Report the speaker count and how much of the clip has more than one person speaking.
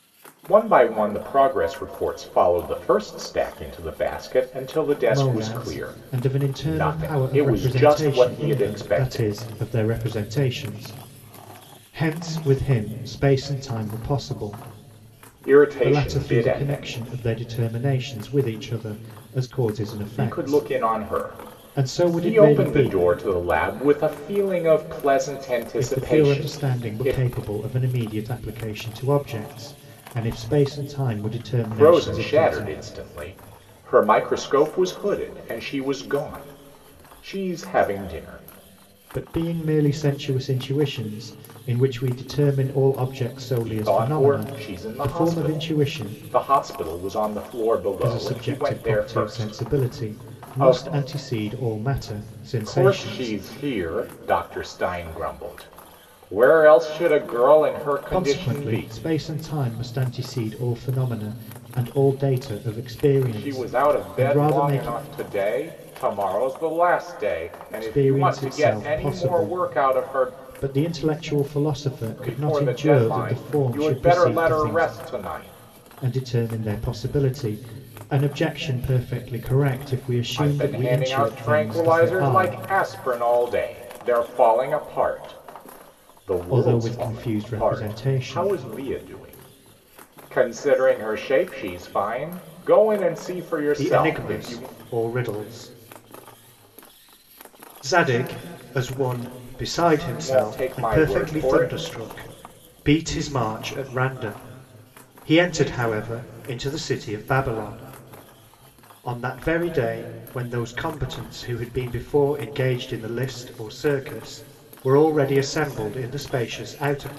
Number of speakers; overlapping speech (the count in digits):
2, about 27%